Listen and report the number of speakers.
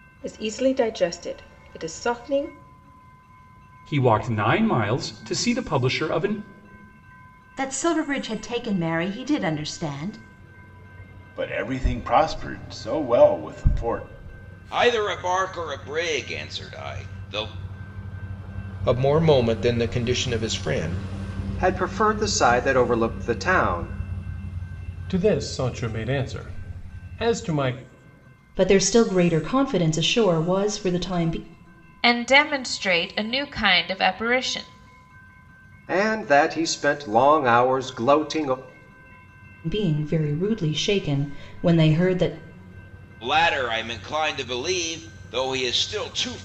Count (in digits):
10